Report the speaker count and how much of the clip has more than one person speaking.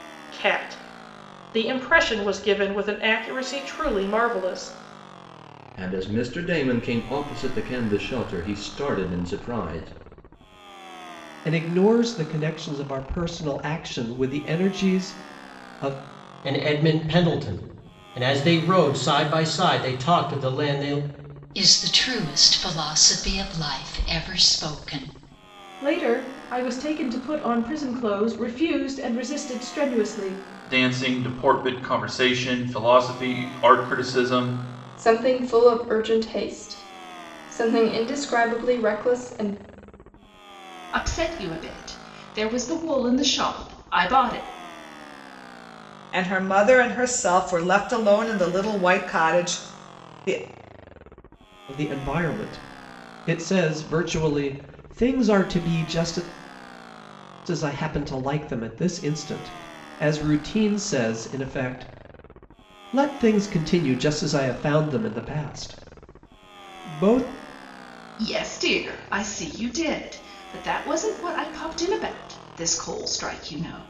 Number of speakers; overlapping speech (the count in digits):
10, no overlap